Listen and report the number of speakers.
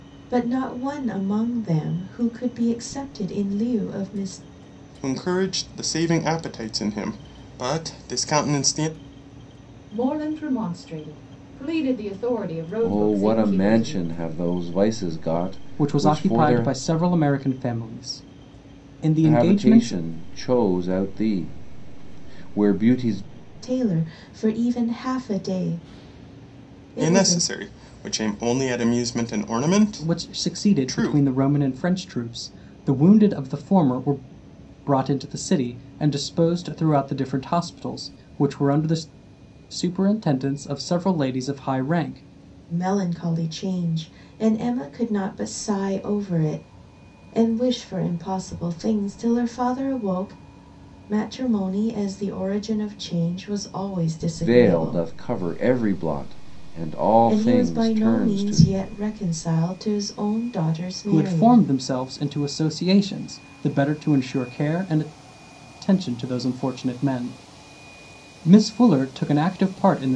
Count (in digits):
5